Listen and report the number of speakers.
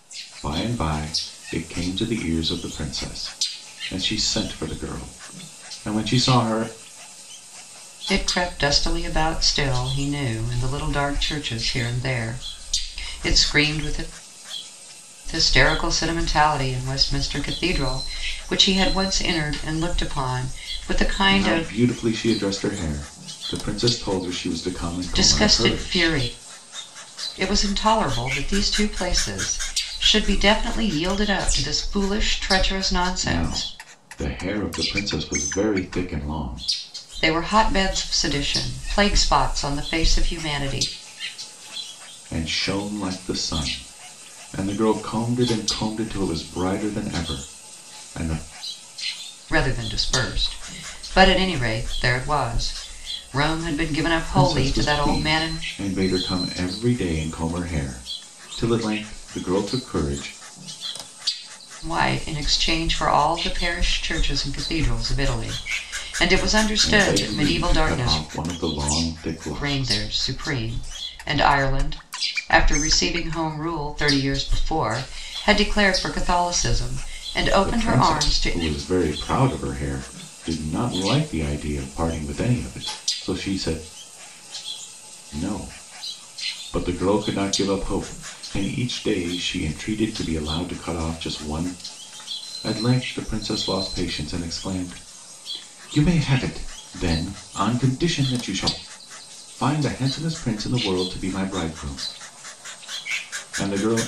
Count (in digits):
2